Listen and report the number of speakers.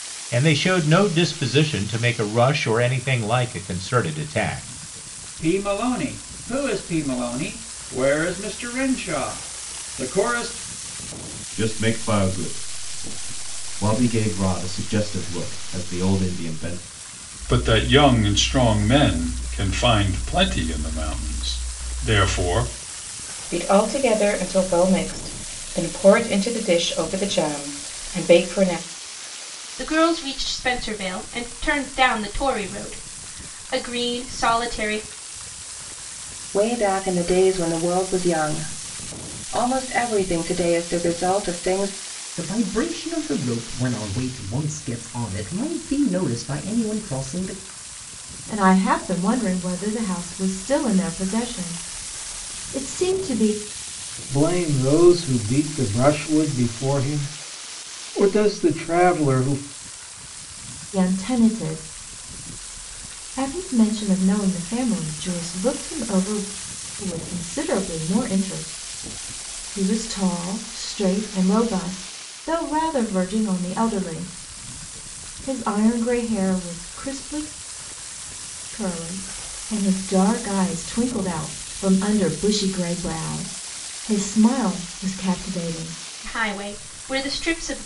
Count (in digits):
10